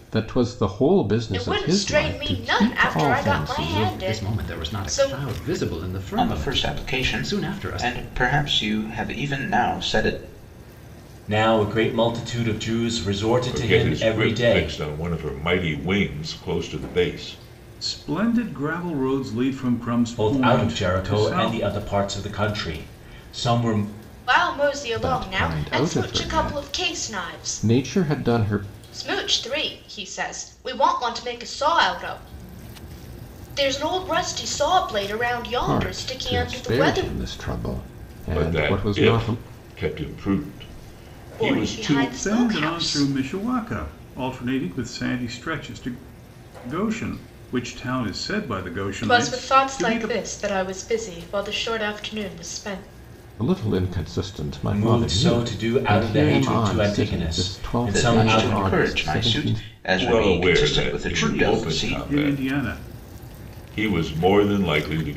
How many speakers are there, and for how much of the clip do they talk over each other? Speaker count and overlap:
7, about 37%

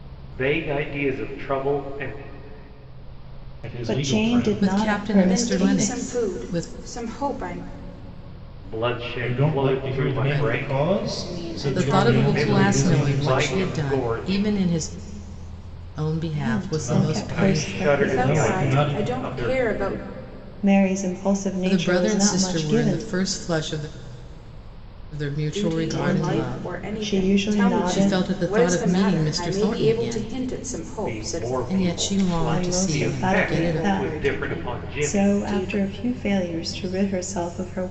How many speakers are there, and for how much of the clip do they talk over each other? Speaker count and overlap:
5, about 60%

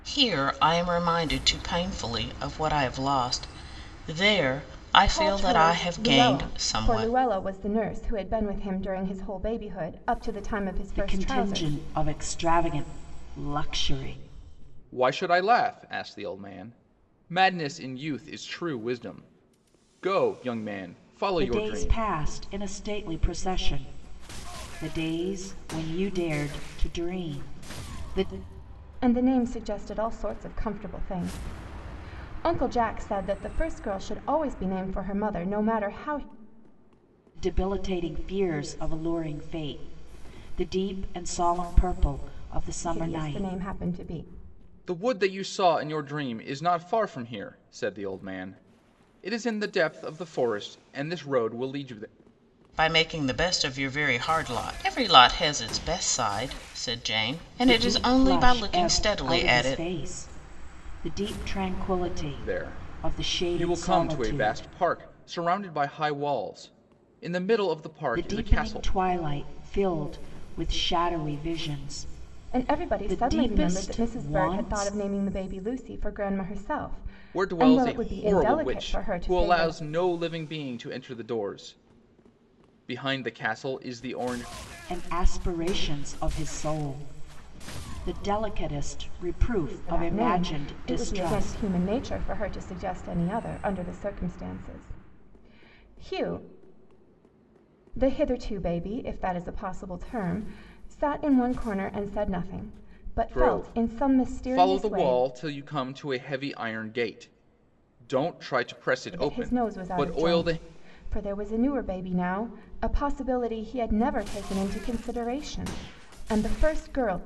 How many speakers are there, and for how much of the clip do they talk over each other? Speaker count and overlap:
4, about 17%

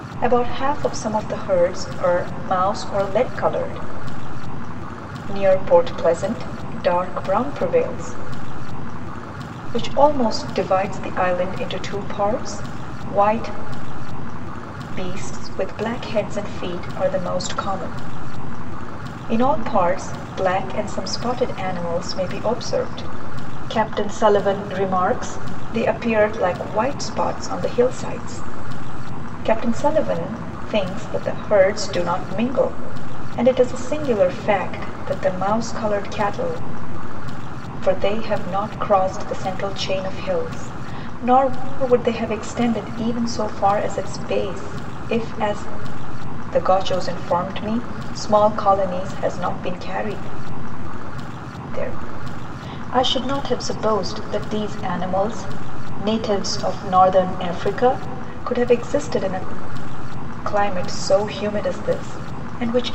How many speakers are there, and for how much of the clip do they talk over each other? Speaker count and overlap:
1, no overlap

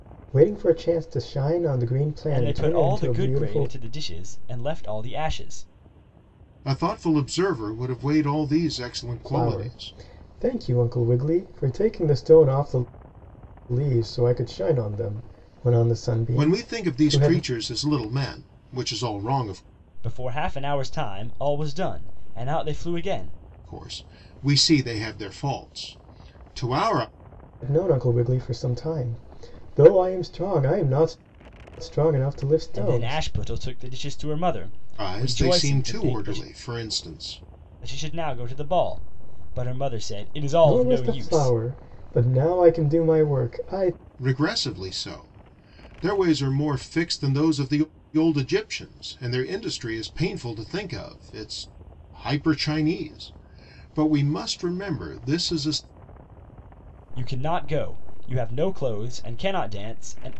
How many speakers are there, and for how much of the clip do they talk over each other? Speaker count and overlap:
3, about 10%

